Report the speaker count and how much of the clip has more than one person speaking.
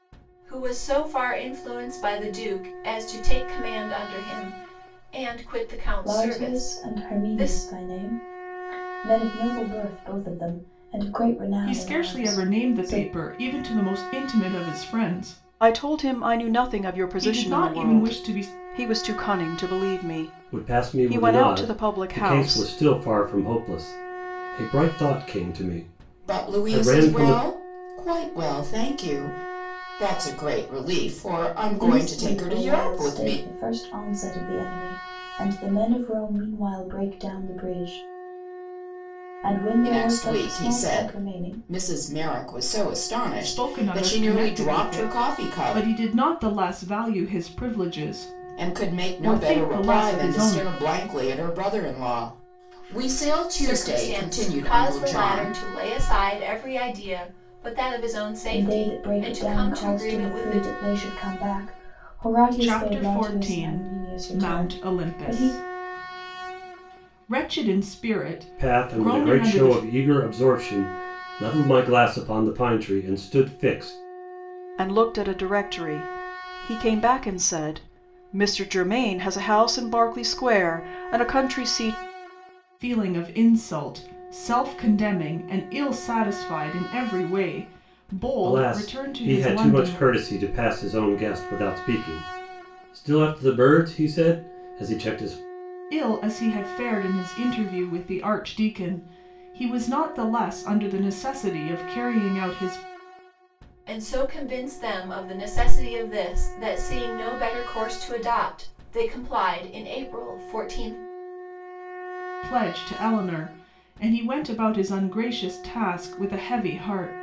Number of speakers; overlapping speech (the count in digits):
6, about 24%